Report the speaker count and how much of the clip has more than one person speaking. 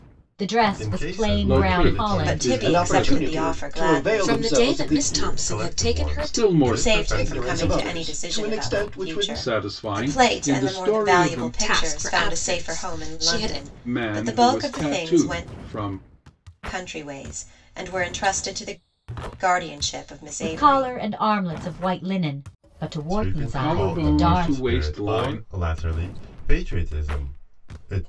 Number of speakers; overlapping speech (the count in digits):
6, about 62%